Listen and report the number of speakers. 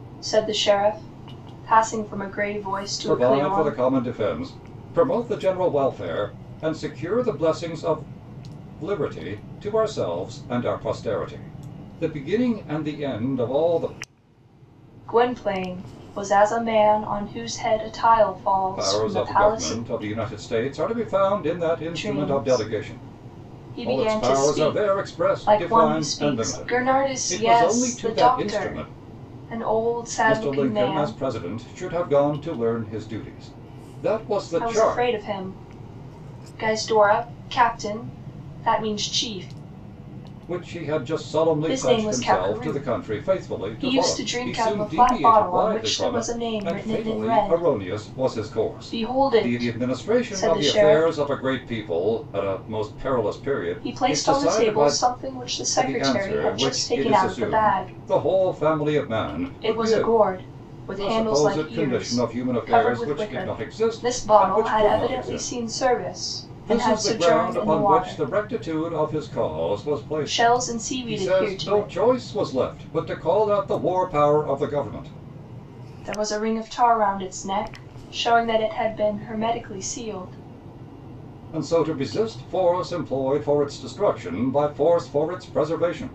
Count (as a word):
two